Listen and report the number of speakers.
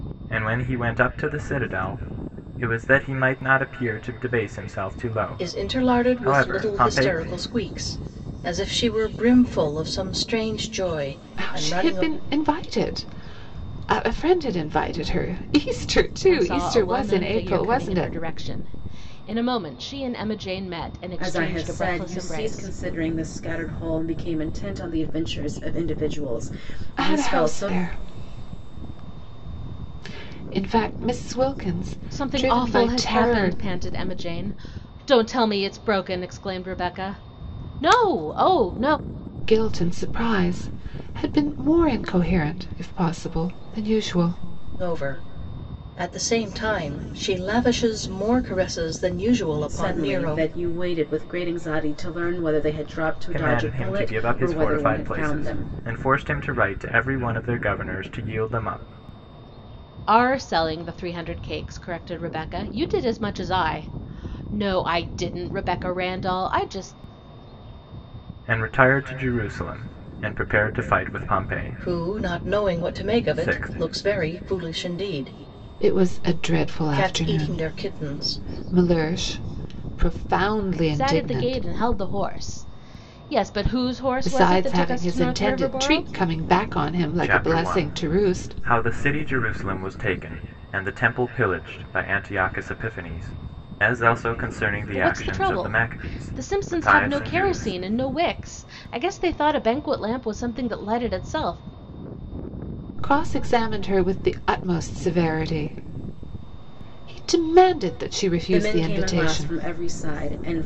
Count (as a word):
five